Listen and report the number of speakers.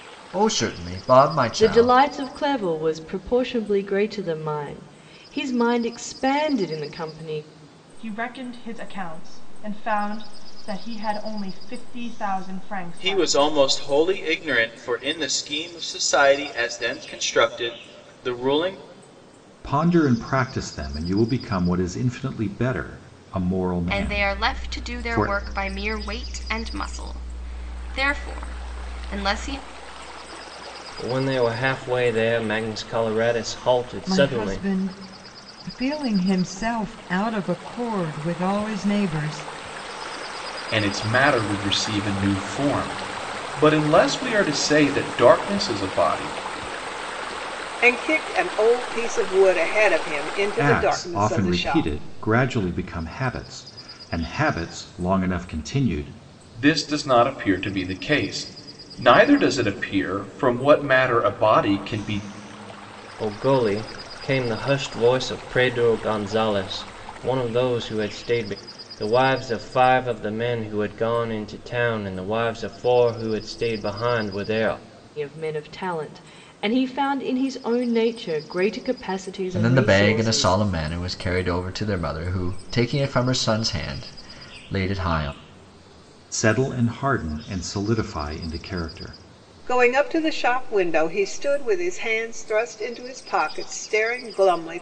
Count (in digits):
10